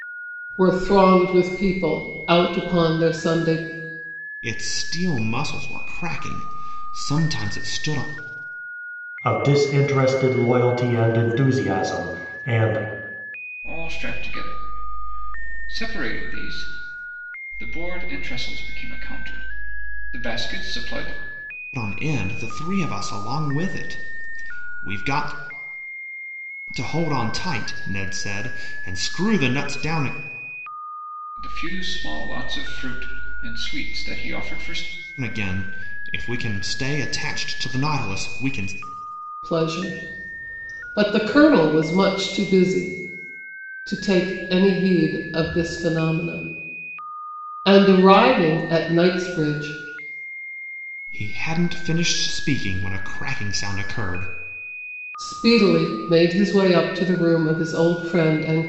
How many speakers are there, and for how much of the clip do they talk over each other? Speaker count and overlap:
four, no overlap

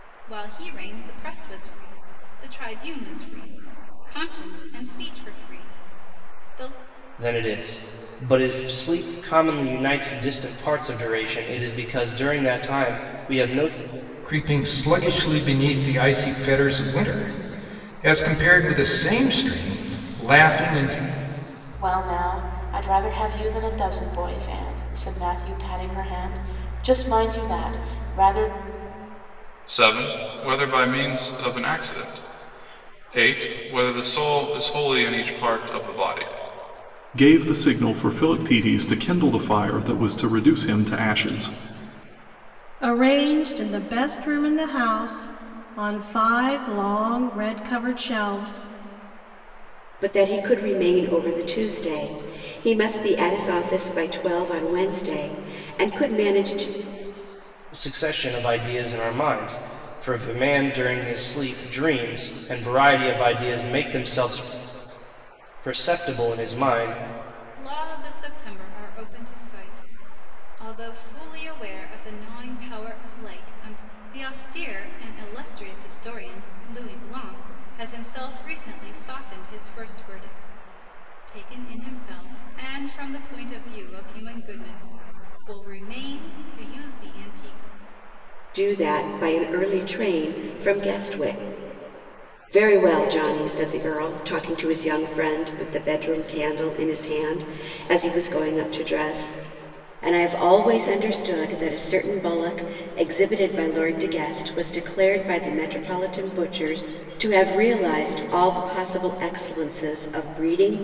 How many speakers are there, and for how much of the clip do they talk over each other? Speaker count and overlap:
eight, no overlap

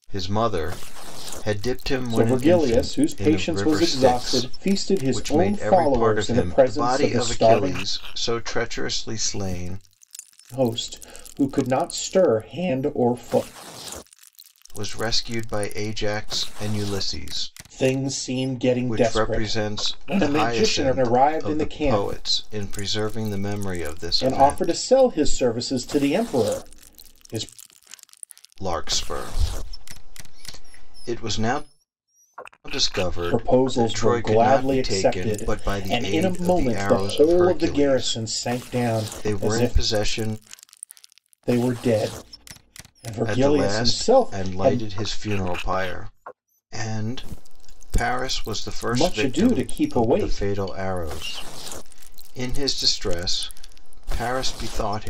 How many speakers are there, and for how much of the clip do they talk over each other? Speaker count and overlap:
two, about 34%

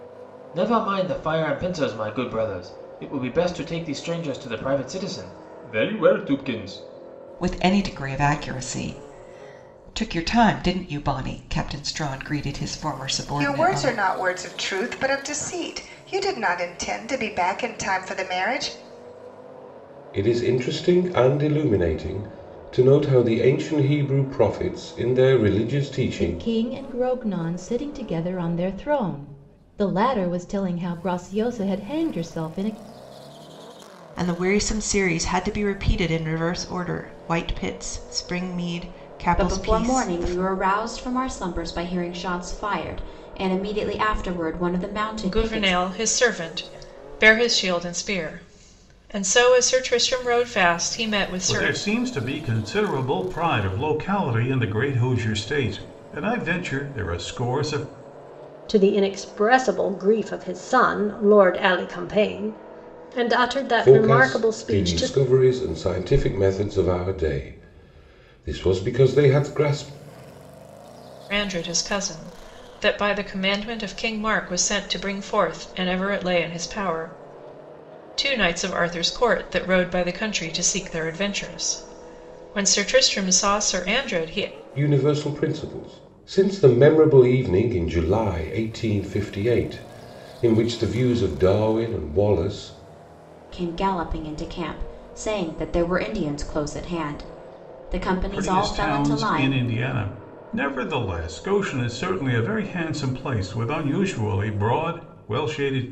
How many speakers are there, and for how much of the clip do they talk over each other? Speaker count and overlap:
ten, about 5%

